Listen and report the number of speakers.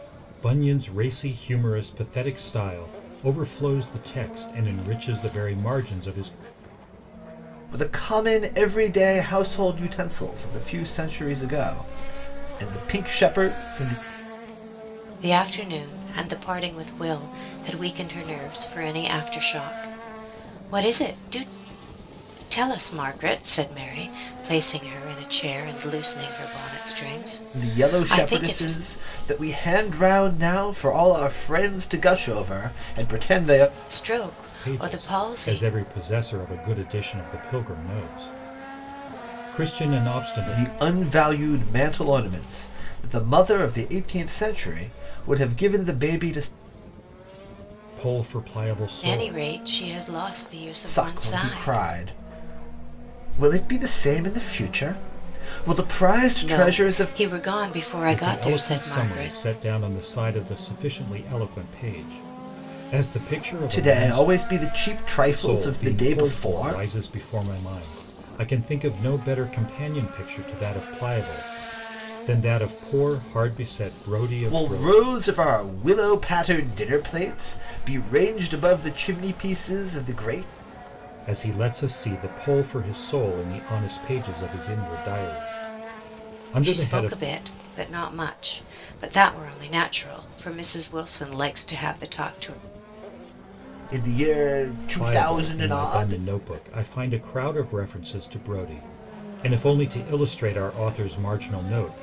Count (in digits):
3